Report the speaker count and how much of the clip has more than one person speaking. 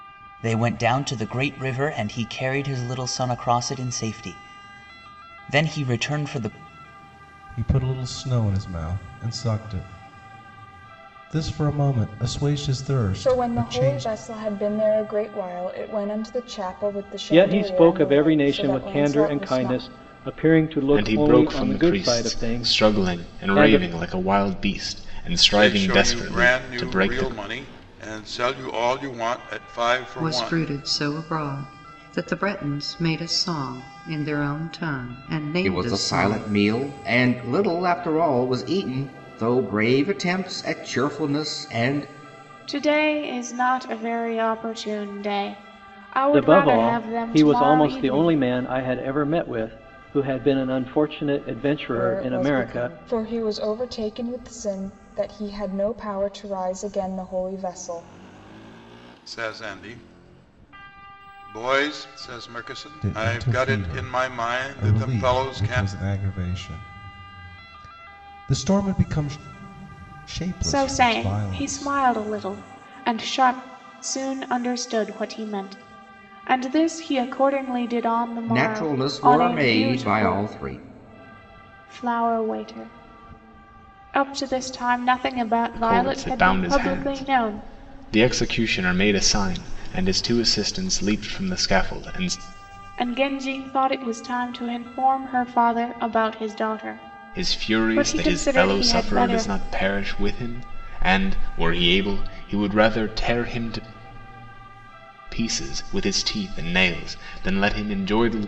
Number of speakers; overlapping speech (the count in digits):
9, about 22%